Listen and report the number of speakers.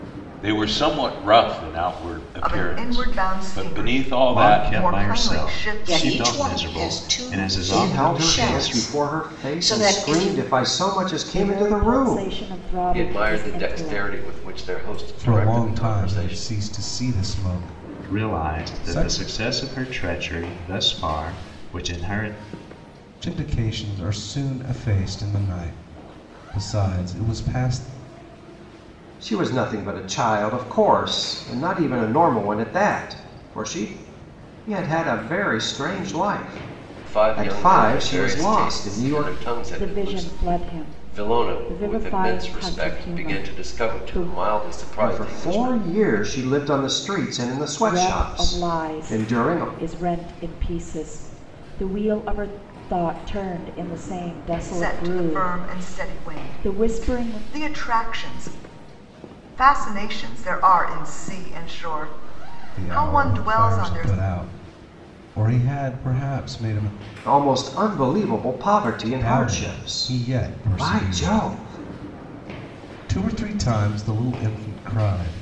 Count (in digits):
8